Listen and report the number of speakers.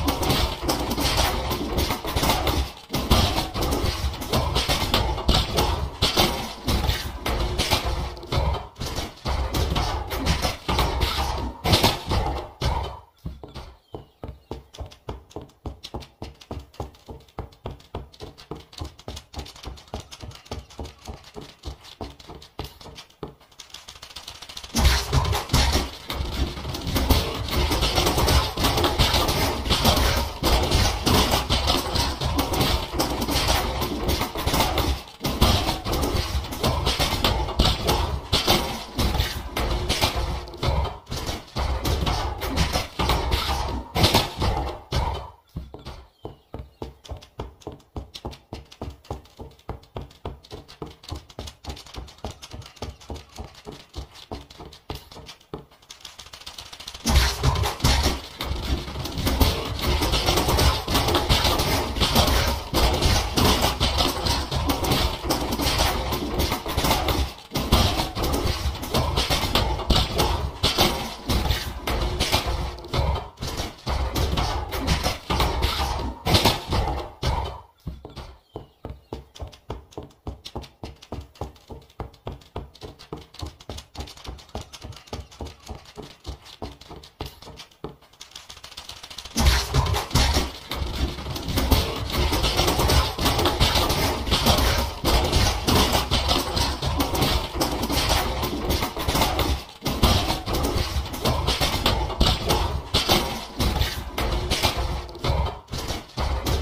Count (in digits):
0